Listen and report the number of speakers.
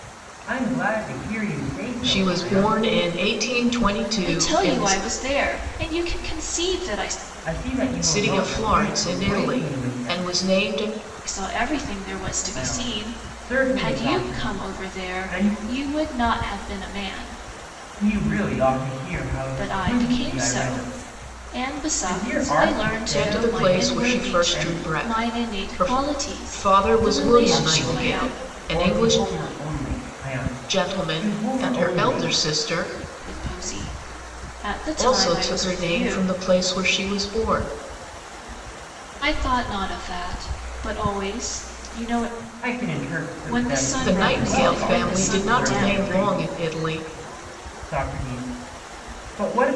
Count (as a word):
three